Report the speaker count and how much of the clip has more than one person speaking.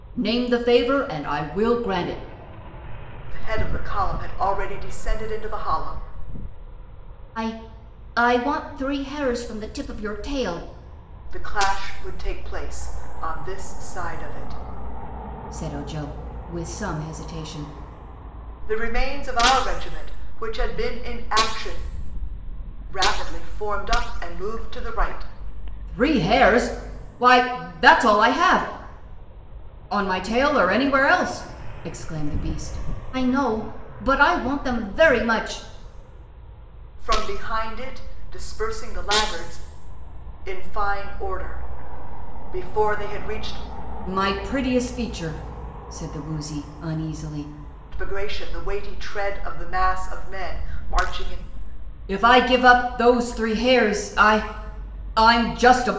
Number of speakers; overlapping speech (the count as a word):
two, no overlap